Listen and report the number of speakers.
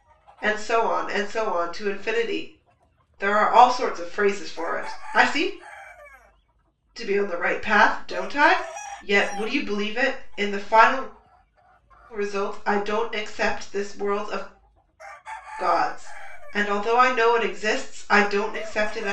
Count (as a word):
one